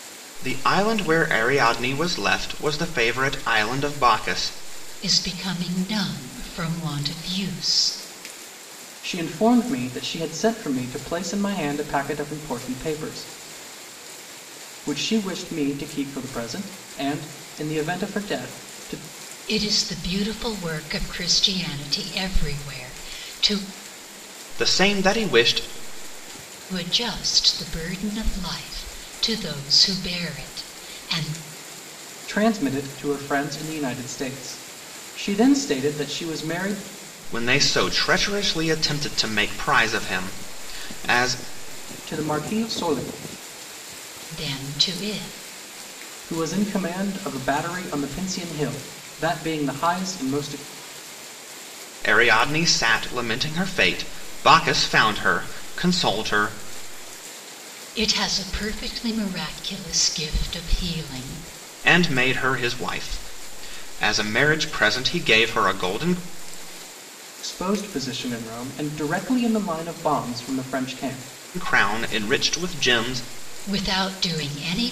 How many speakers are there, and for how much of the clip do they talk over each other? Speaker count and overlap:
3, no overlap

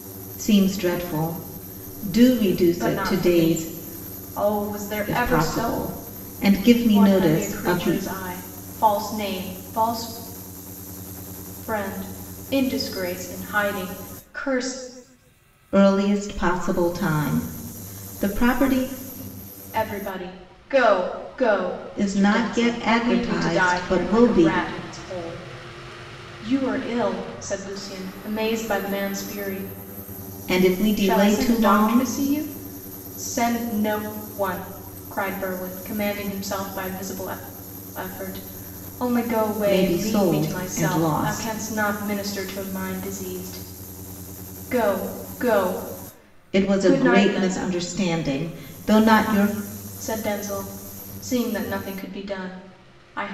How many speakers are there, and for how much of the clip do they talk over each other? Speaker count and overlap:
2, about 18%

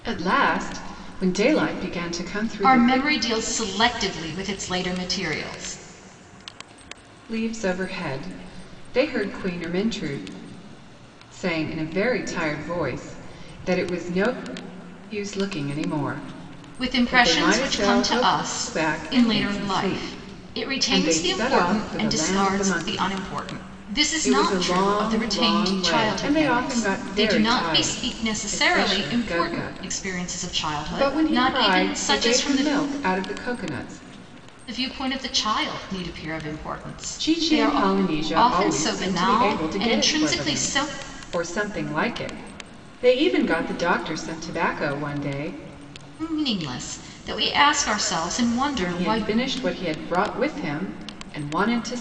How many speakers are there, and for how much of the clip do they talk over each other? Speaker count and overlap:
2, about 35%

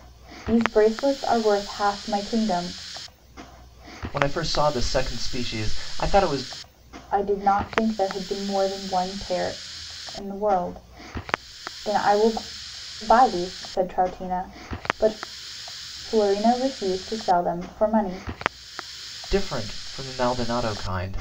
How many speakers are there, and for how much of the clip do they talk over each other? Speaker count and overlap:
2, no overlap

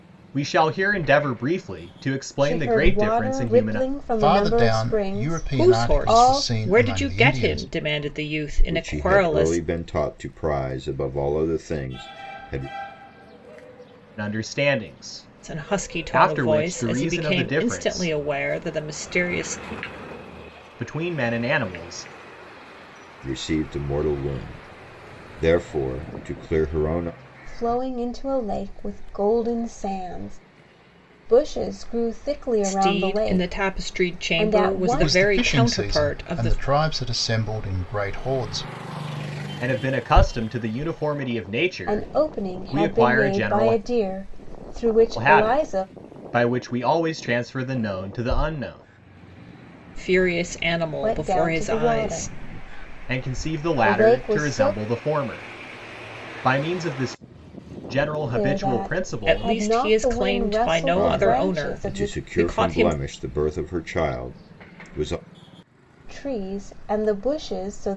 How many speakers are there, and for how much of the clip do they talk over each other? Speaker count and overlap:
5, about 34%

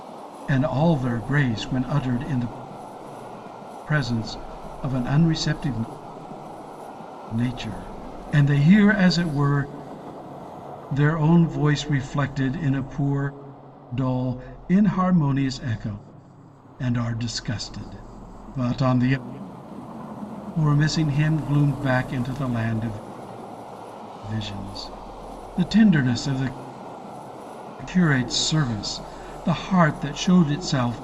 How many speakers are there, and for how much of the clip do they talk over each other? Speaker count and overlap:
1, no overlap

